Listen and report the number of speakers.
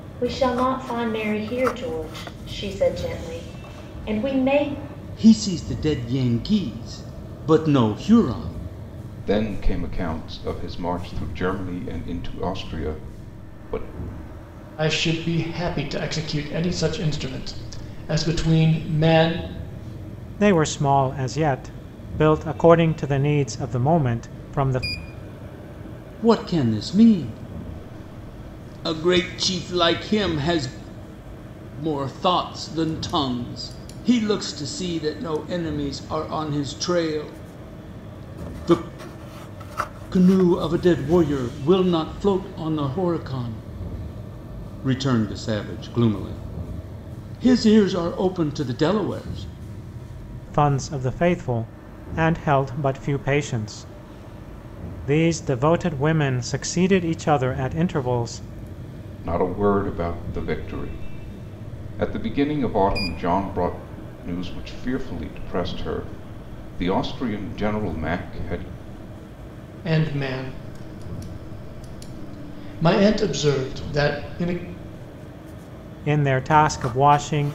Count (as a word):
five